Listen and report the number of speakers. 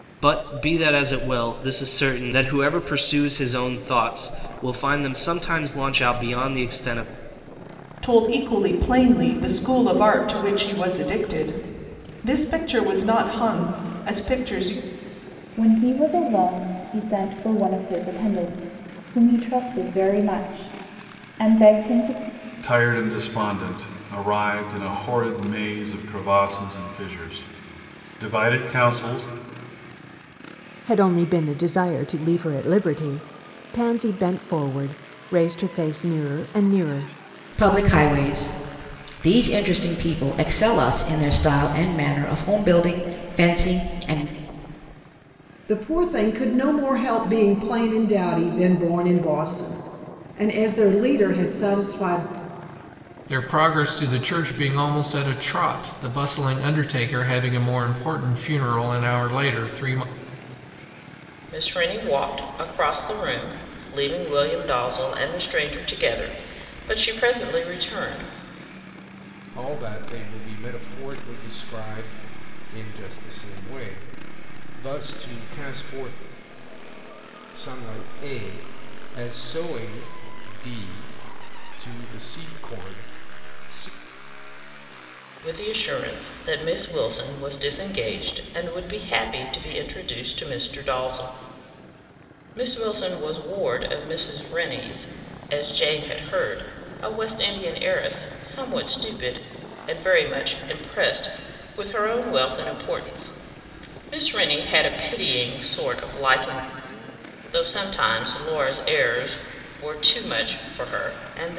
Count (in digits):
10